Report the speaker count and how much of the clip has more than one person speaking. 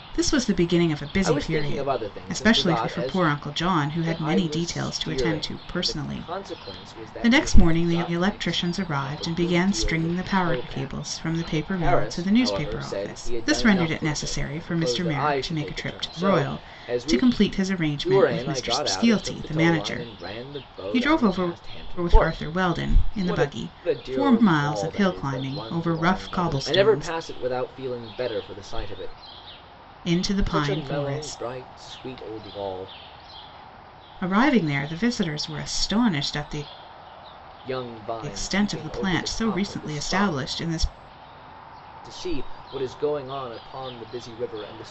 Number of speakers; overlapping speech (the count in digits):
2, about 57%